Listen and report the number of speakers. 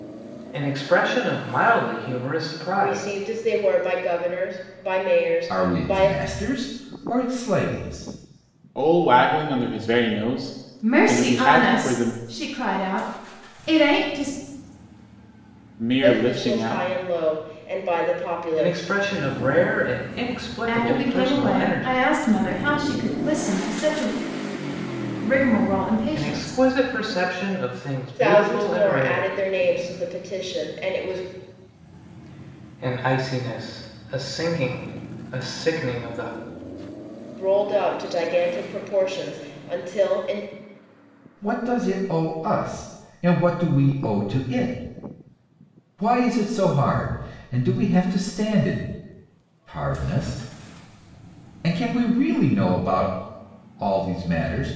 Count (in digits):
5